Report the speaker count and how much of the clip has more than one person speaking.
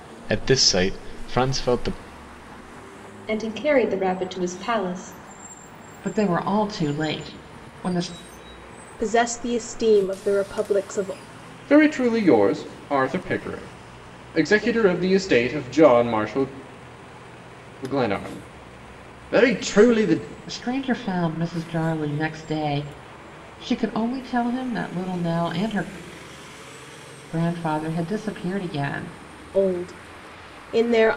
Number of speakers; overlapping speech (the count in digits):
5, no overlap